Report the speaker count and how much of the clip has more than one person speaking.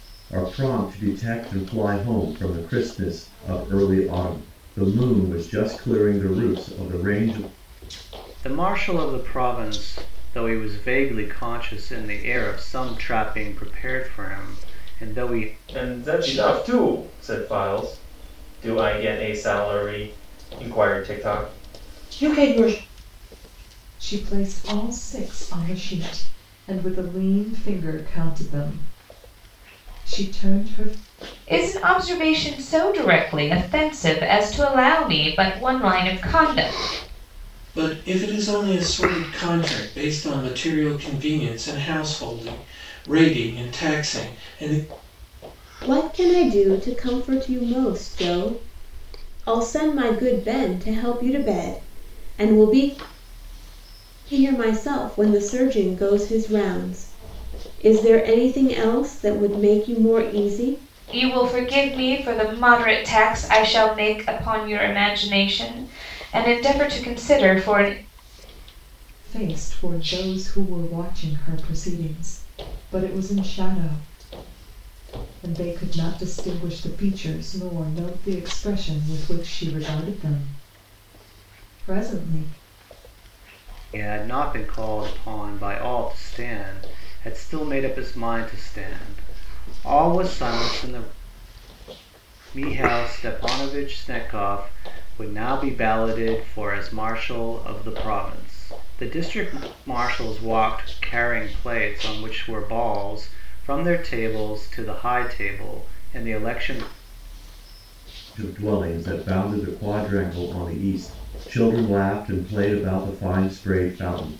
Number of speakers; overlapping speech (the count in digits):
7, no overlap